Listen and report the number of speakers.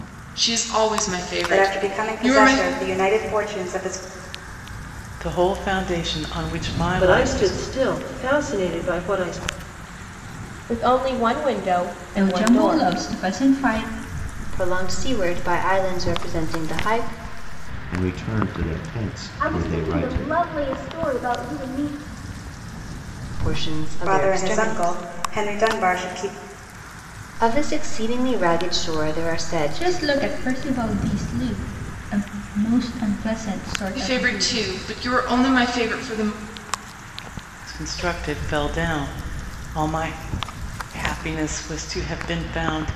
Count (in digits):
9